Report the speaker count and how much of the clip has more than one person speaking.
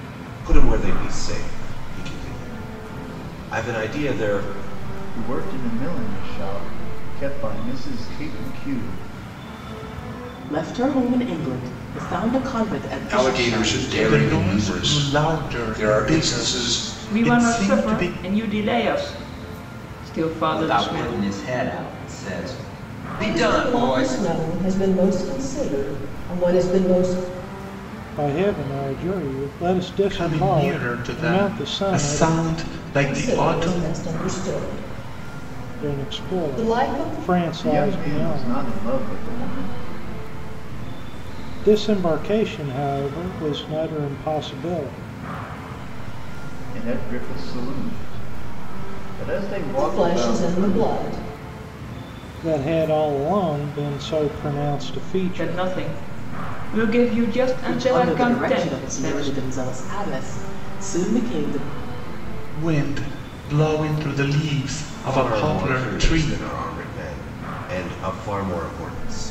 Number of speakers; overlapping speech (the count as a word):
ten, about 44%